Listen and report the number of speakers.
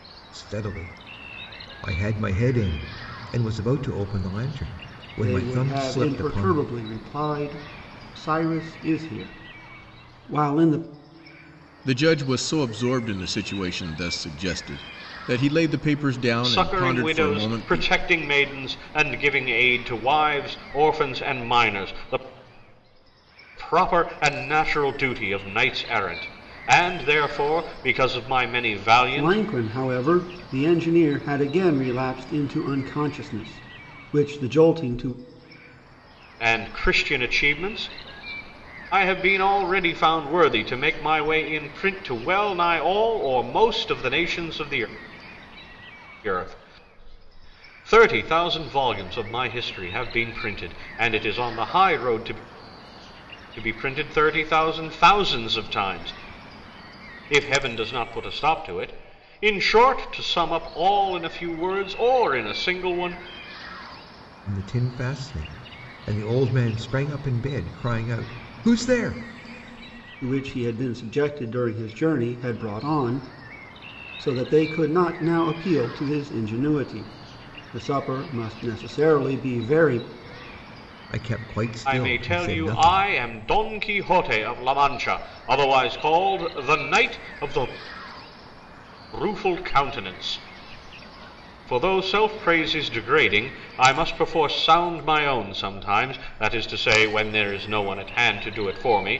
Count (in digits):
4